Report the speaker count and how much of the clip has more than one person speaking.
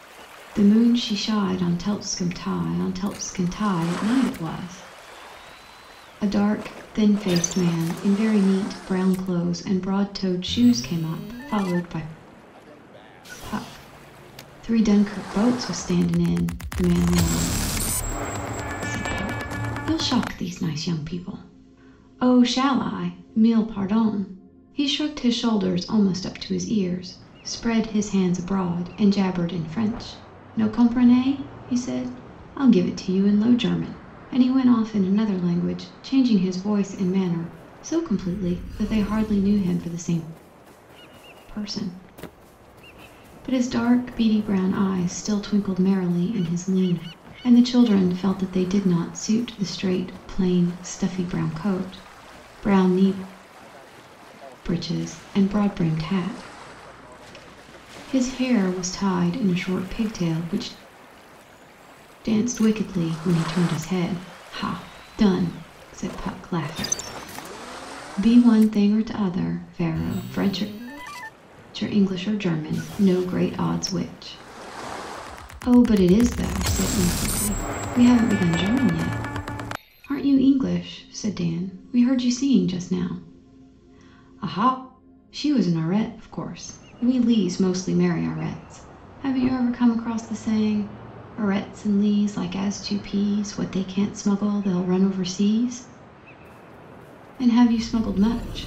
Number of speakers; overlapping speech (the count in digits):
1, no overlap